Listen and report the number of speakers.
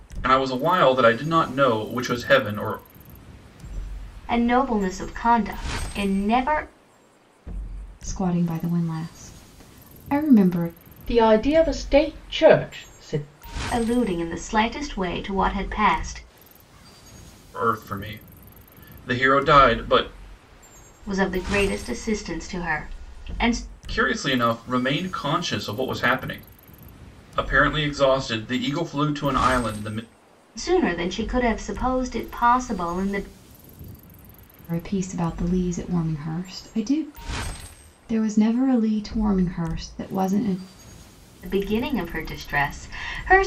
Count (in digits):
4